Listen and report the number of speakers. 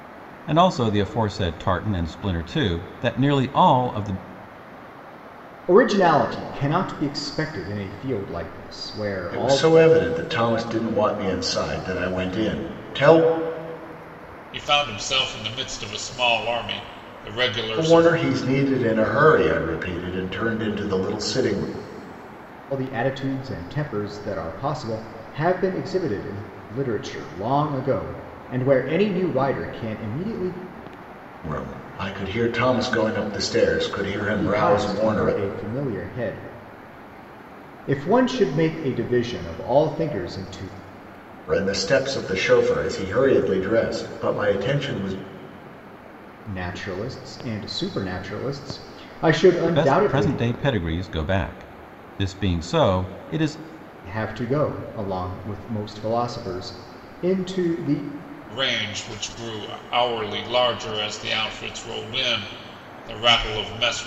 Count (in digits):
4